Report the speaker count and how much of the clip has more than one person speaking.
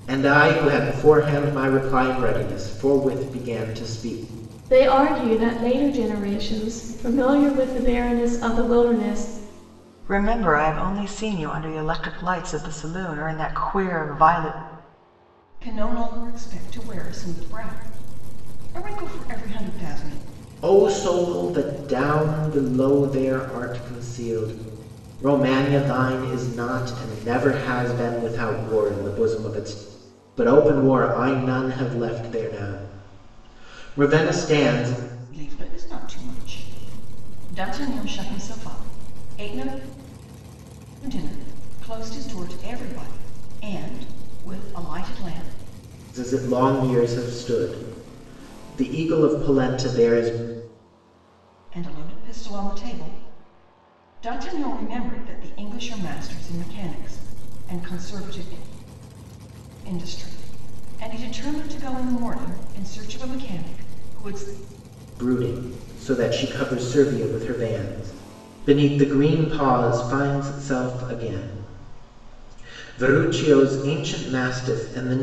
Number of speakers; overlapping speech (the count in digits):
4, no overlap